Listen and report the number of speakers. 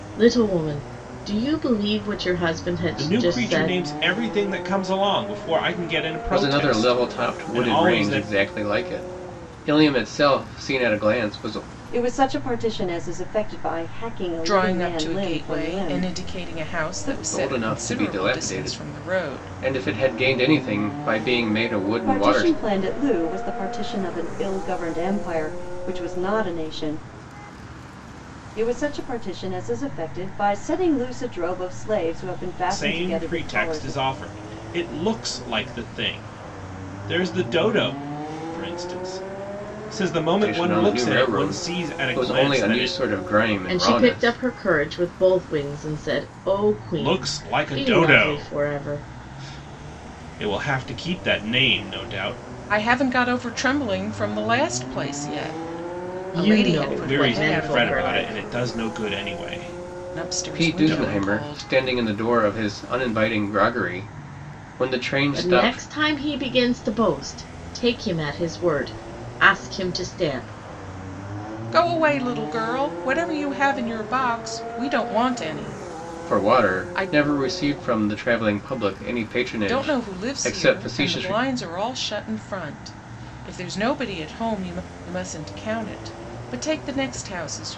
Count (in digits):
5